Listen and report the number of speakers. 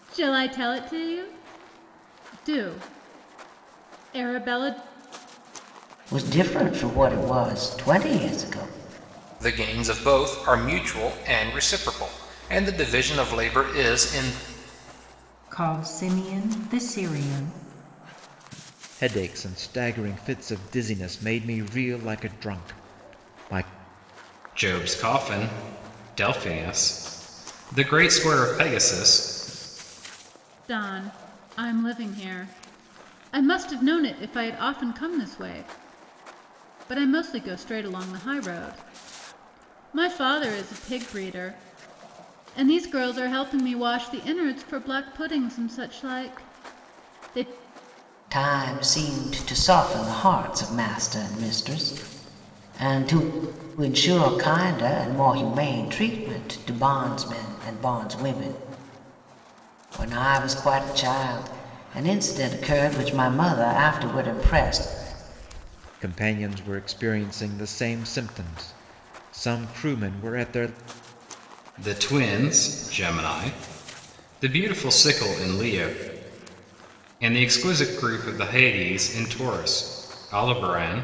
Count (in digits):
6